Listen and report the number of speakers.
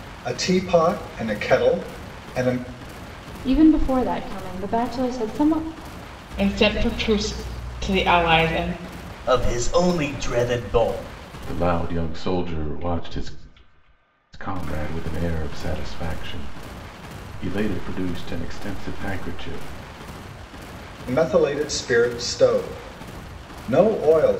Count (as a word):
five